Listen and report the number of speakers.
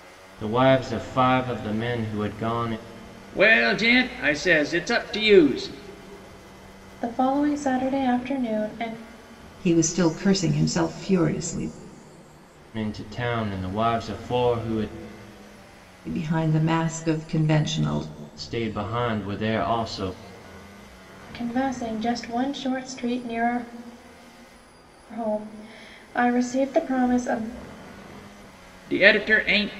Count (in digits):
4